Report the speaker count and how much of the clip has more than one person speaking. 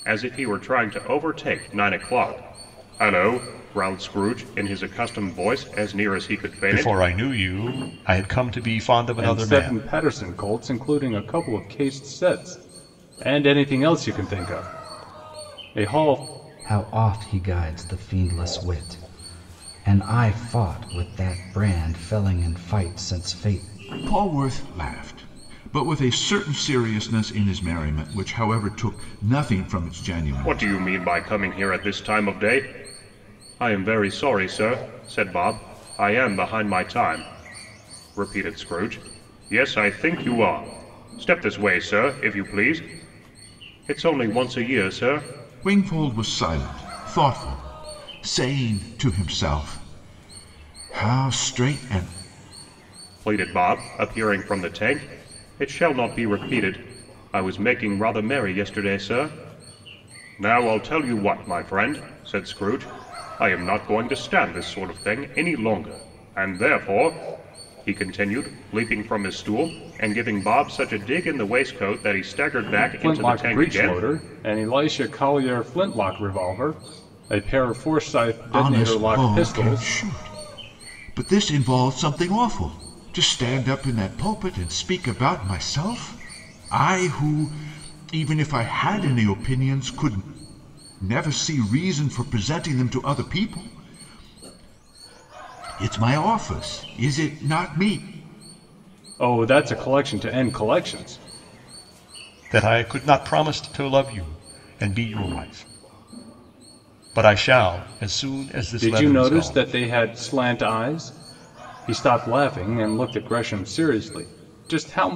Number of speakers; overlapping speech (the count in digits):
5, about 4%